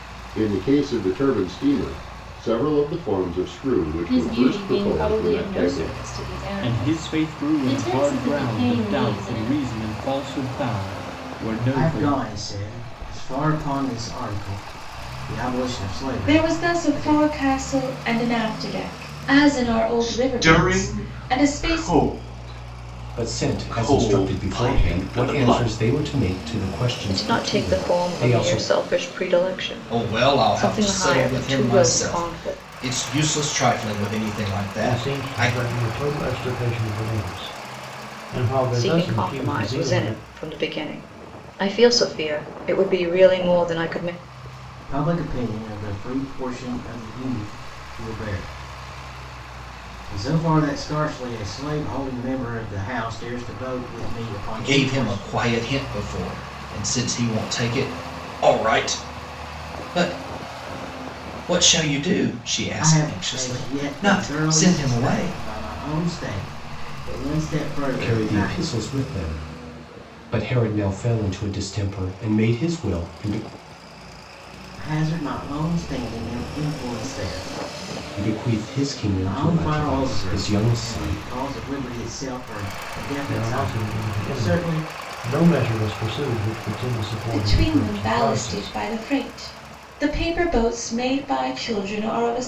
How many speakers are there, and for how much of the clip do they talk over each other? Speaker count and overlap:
ten, about 29%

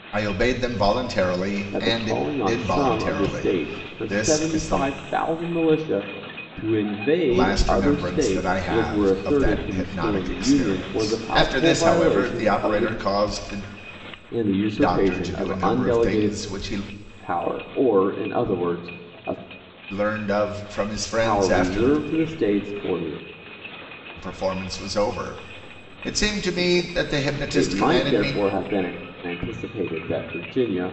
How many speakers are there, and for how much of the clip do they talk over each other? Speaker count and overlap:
two, about 42%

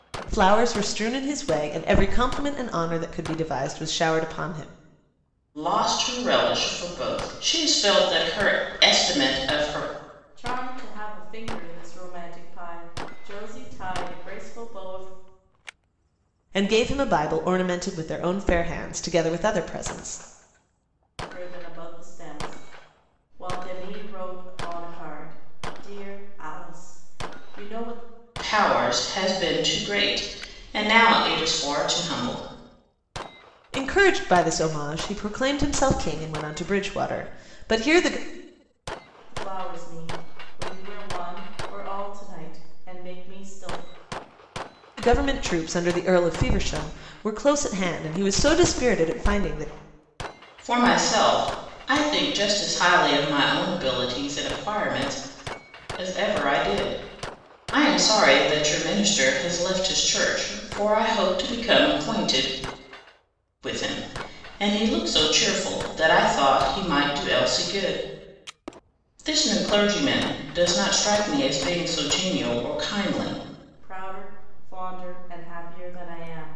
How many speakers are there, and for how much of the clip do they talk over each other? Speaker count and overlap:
three, no overlap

